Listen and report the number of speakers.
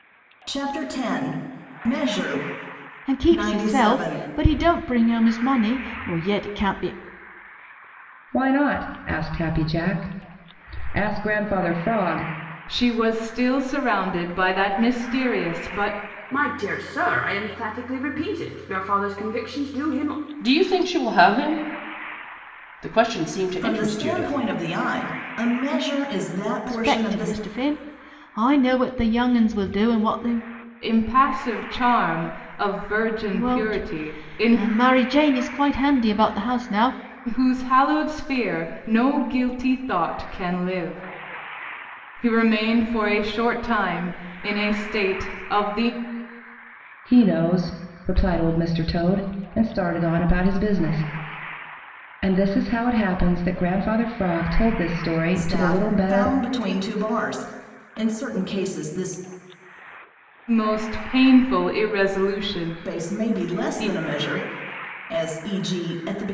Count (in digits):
6